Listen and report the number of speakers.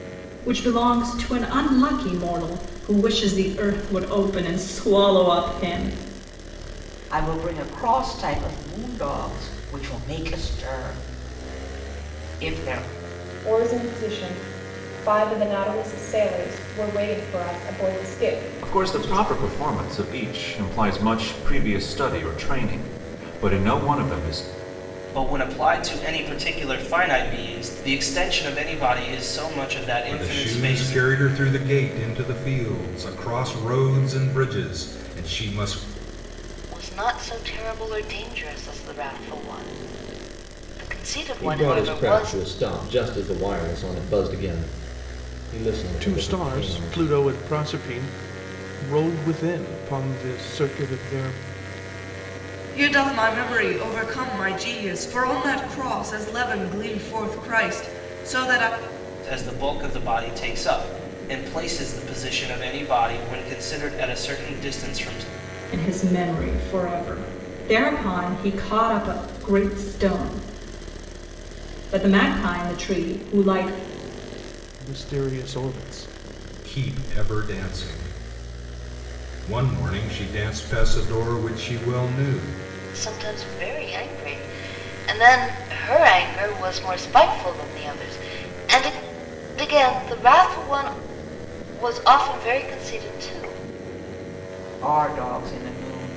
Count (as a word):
ten